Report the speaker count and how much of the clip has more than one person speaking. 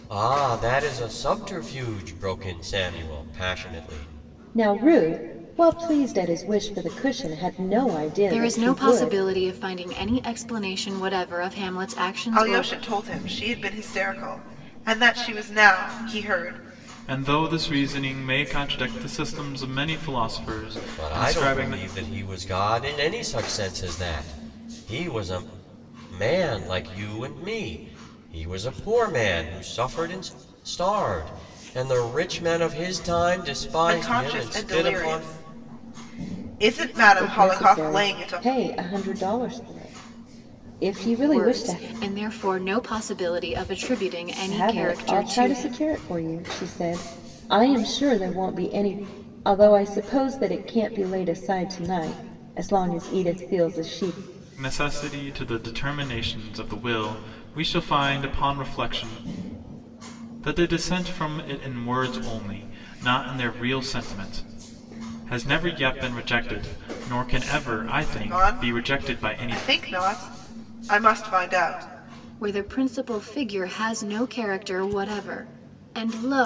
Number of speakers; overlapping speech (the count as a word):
five, about 11%